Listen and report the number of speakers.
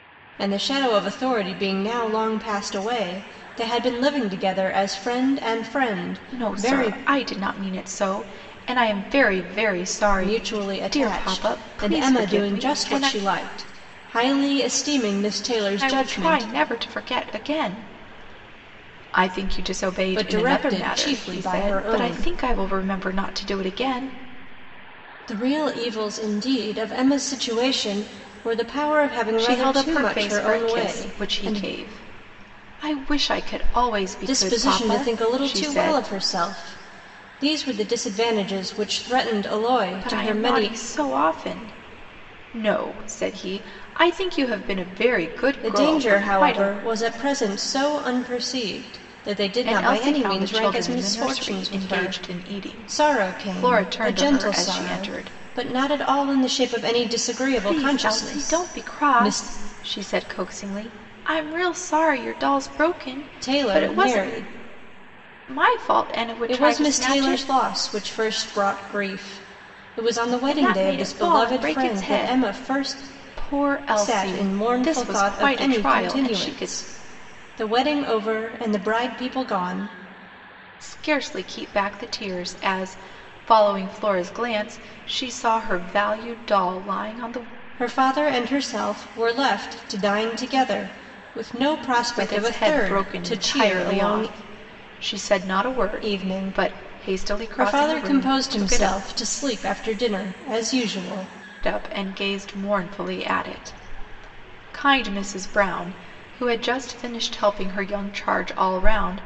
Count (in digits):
2